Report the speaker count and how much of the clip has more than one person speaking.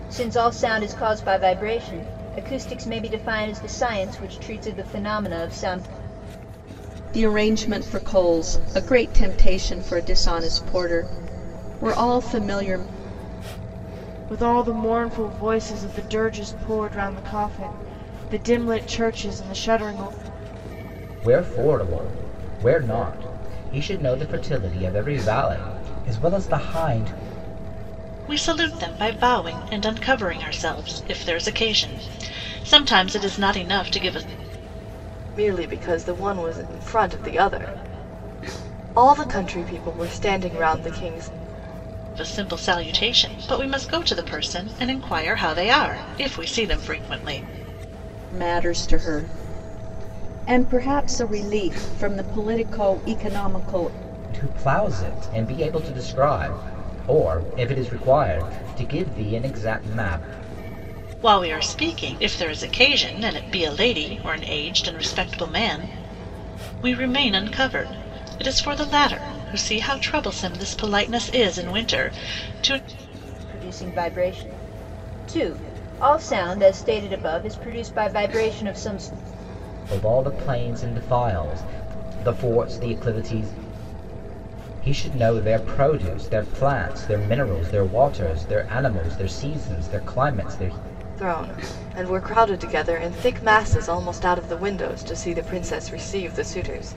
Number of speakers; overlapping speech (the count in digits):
6, no overlap